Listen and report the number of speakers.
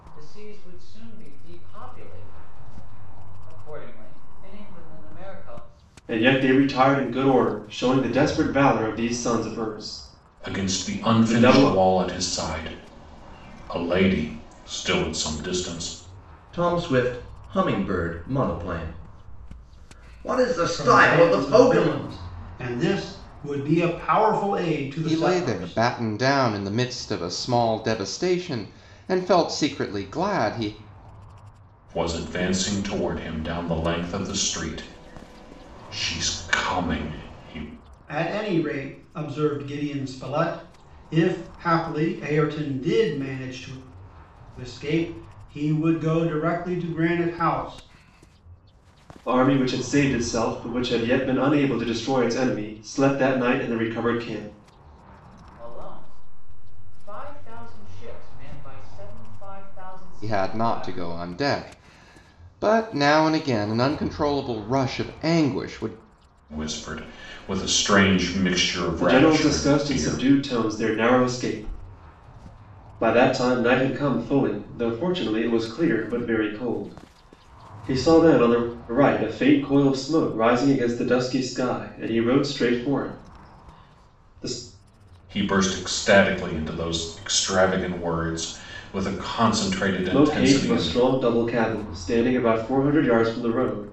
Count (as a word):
six